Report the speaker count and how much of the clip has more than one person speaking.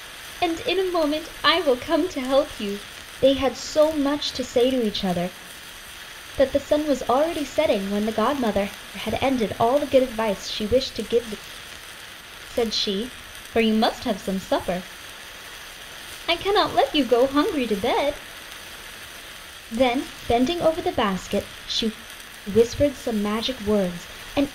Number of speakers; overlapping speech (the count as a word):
one, no overlap